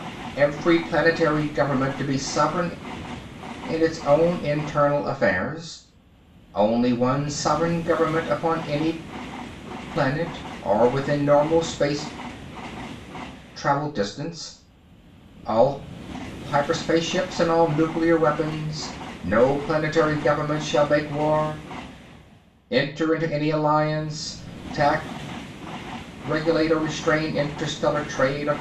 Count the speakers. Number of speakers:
one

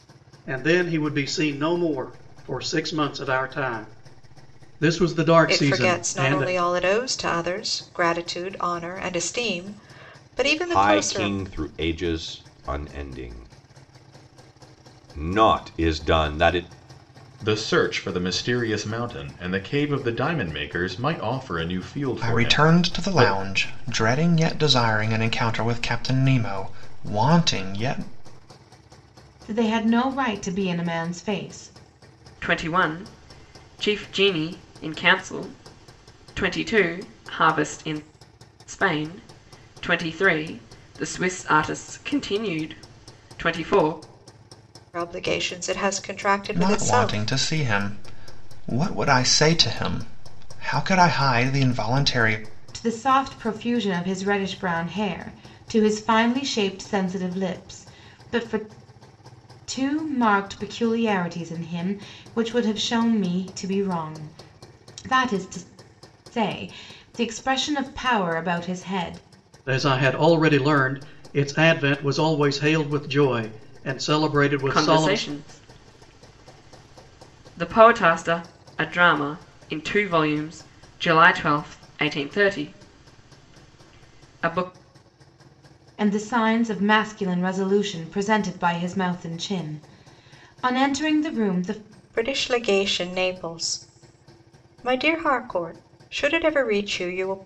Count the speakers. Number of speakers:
seven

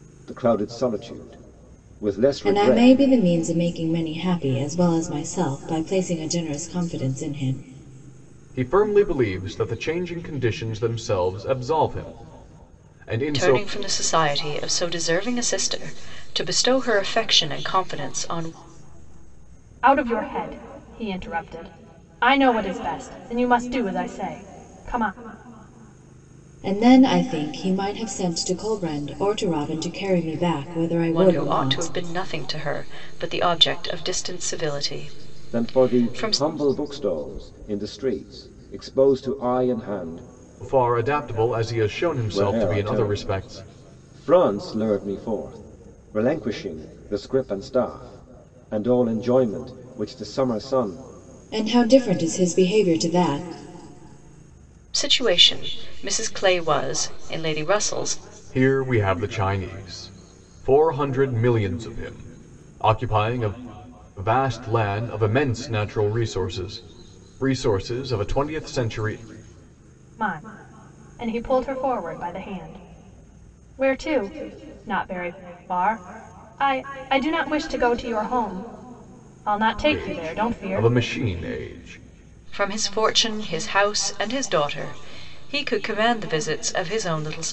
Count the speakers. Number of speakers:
five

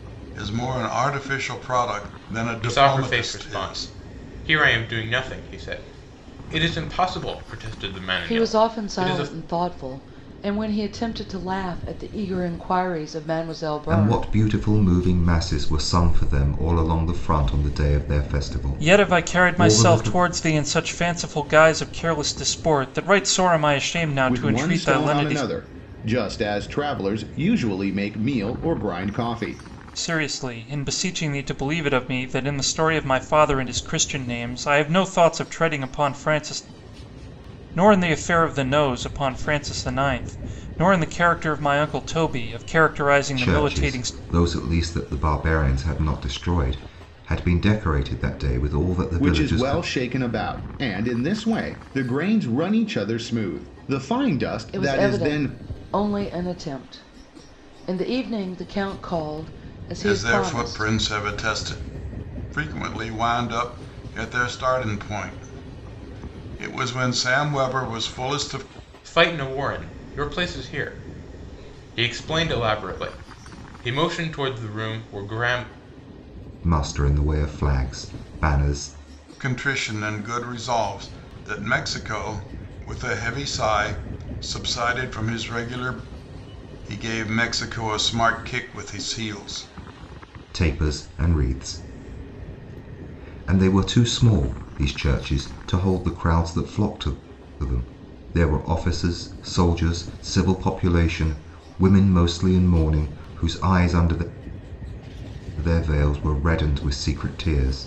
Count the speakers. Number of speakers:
six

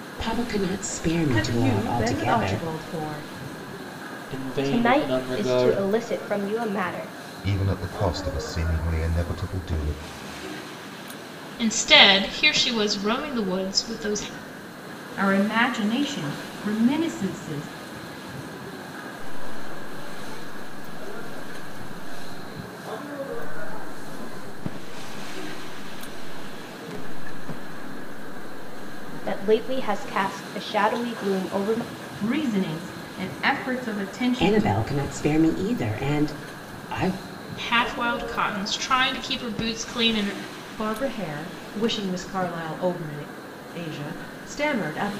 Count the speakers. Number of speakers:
eight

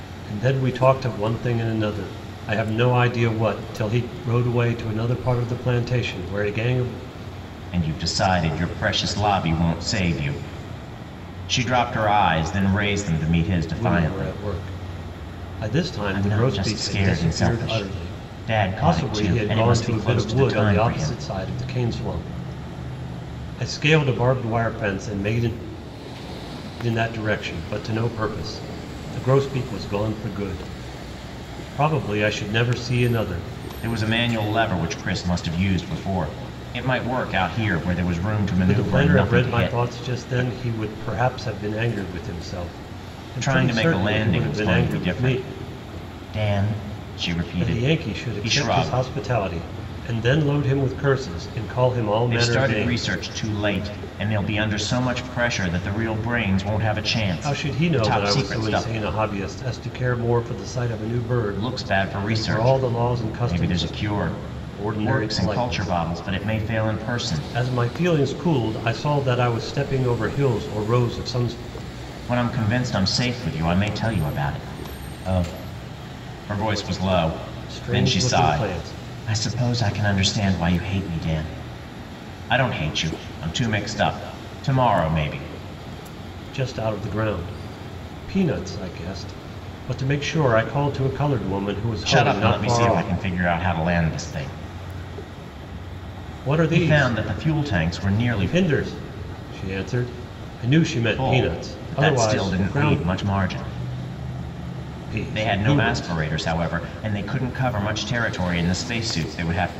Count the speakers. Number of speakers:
two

